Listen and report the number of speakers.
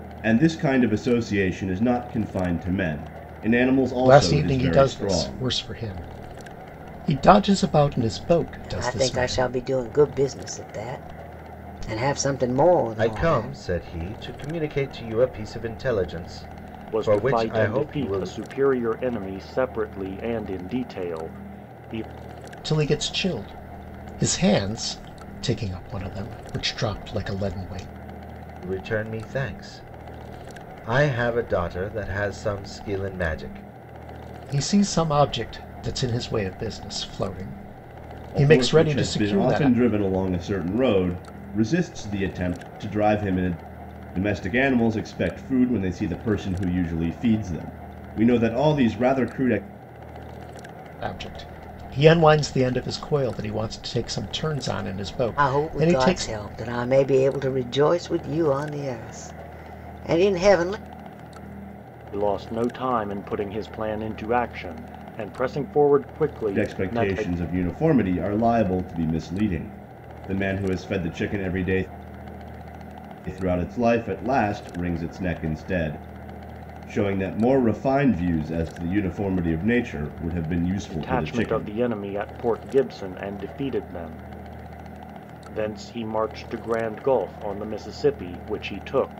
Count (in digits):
5